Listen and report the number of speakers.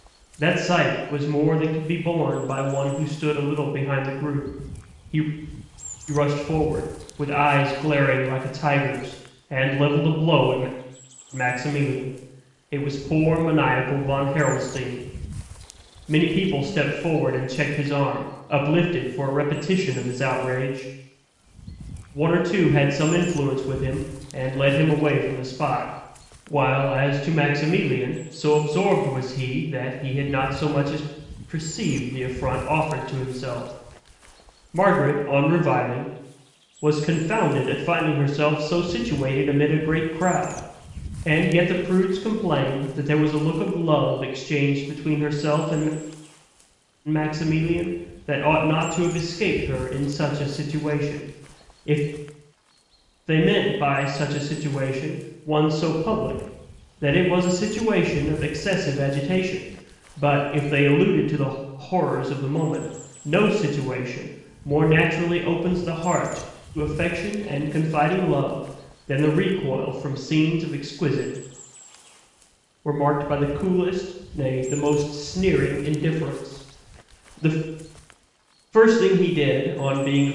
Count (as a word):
one